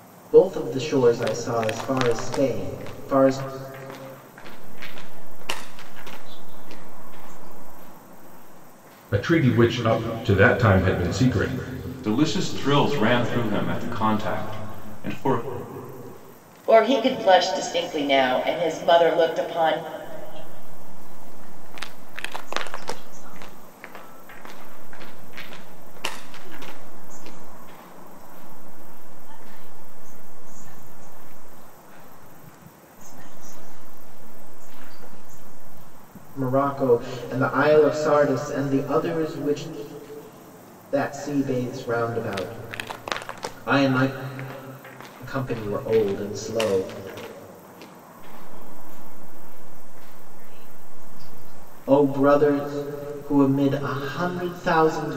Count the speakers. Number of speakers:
5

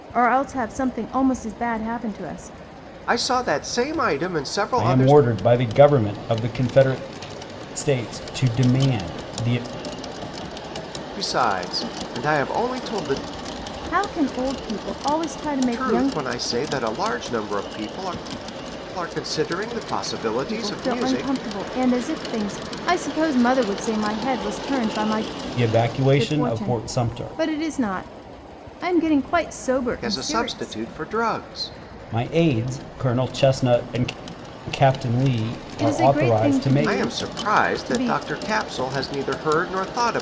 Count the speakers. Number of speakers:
3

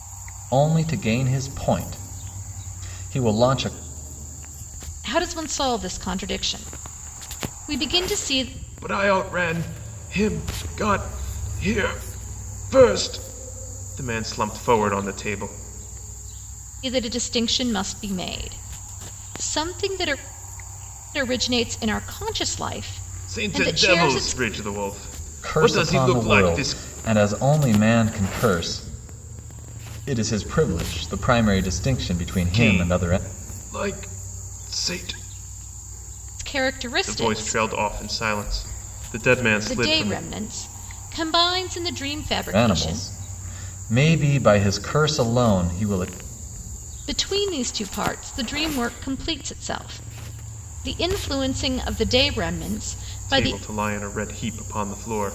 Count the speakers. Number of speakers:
3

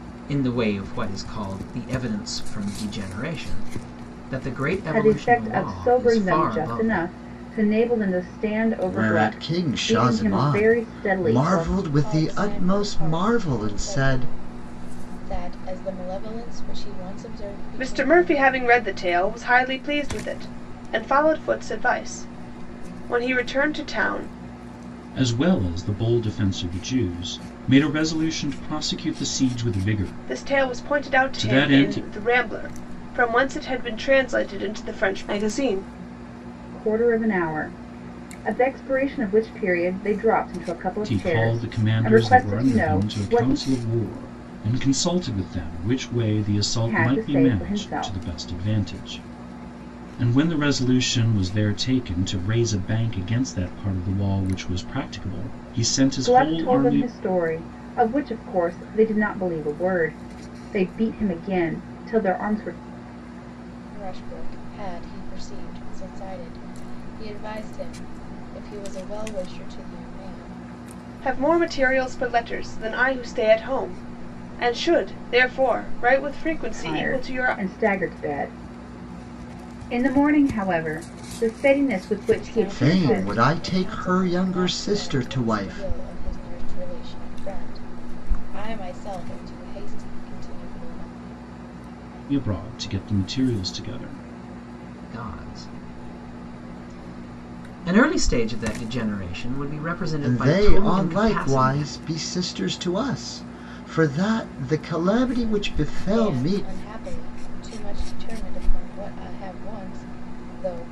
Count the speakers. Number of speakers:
6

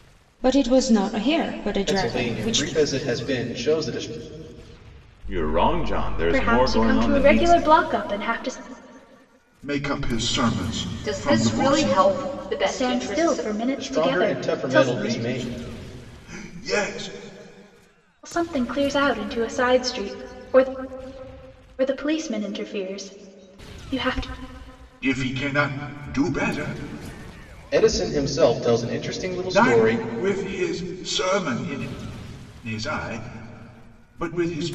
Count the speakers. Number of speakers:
6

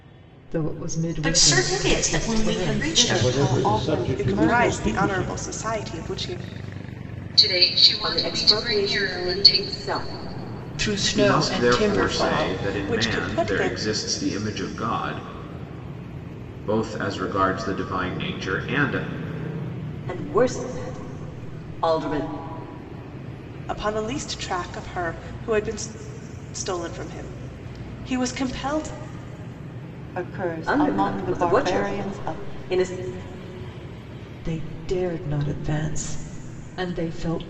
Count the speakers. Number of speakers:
9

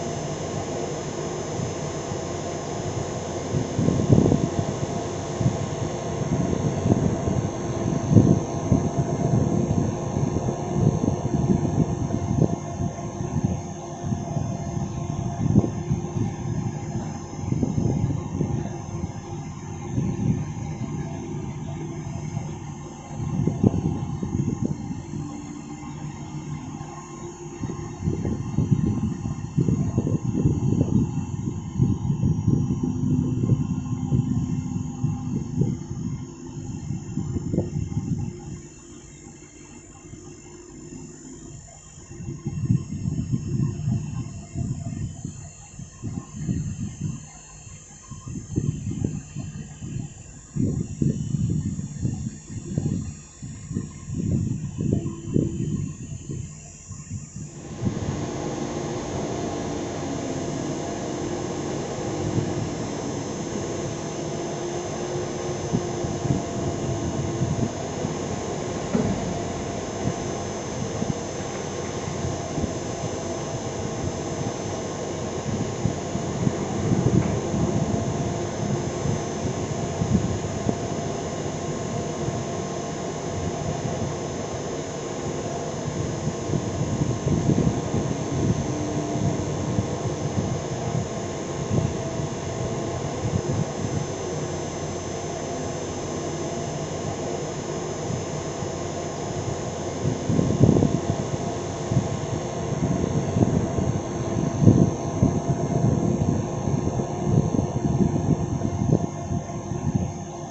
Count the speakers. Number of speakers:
0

